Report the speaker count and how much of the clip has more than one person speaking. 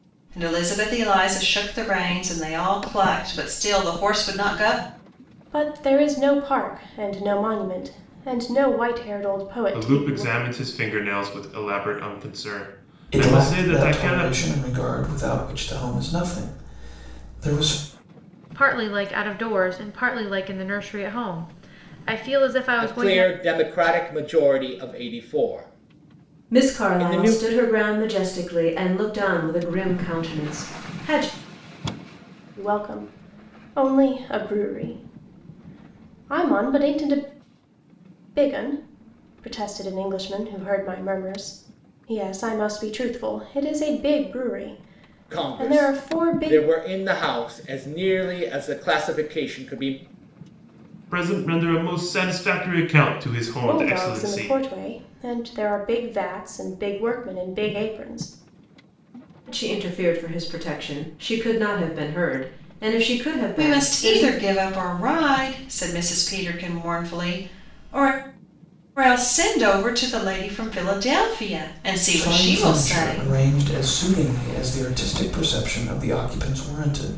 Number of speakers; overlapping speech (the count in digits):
7, about 10%